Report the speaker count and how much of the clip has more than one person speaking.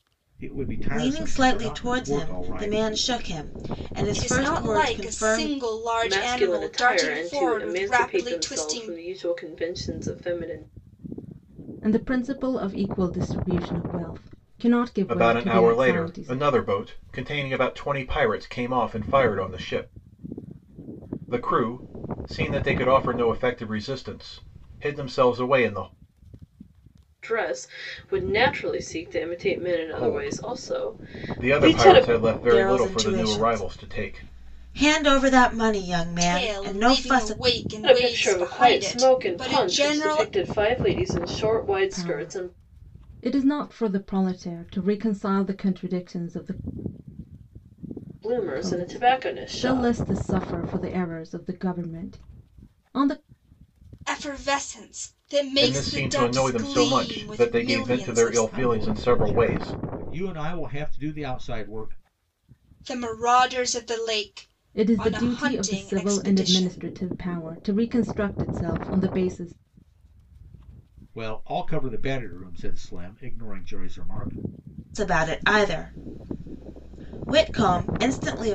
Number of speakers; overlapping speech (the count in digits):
6, about 30%